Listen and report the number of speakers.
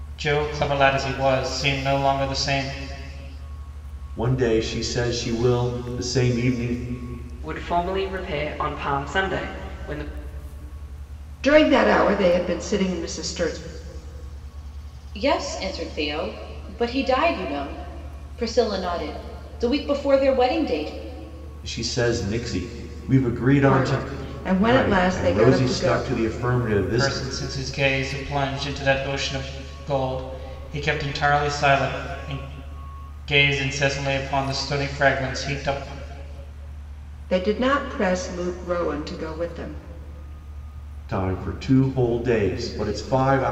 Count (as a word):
five